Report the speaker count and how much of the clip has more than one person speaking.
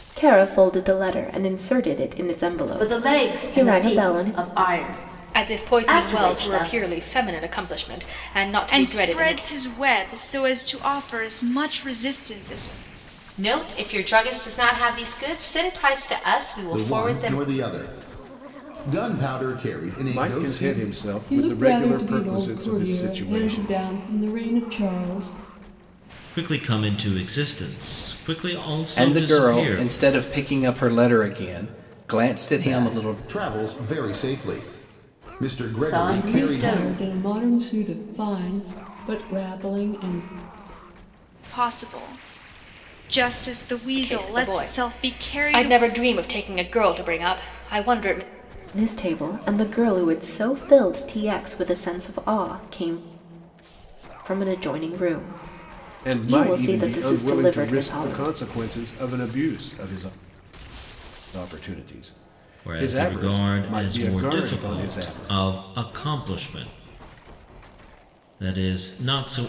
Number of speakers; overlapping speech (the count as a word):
ten, about 26%